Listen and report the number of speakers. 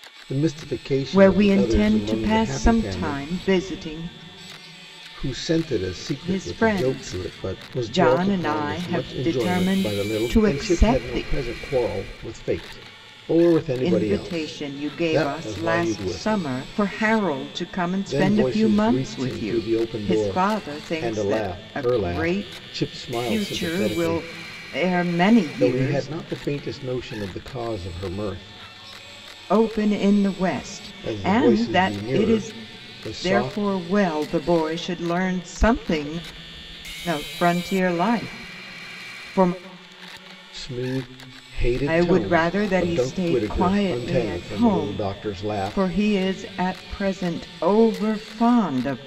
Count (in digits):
2